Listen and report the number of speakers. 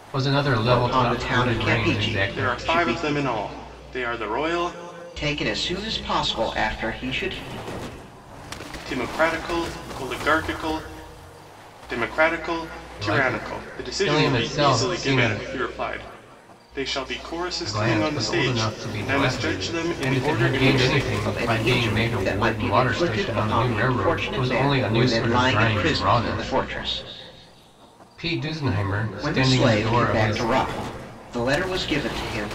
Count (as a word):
three